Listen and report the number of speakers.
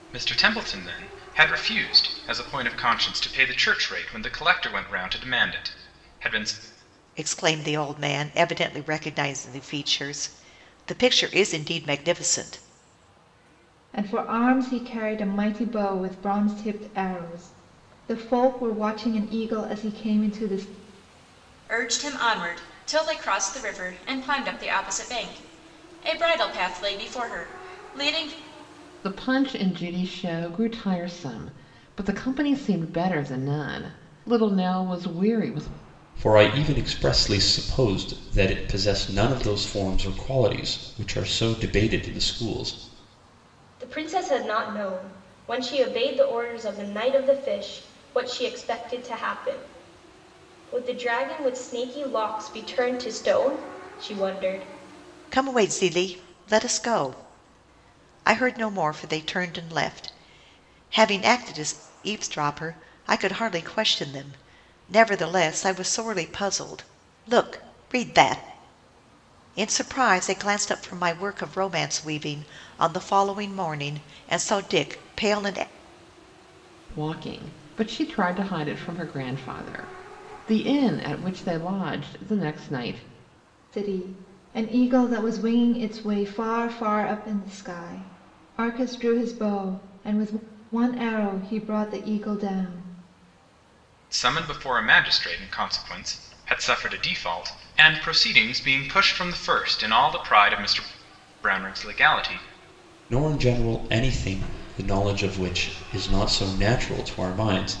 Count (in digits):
7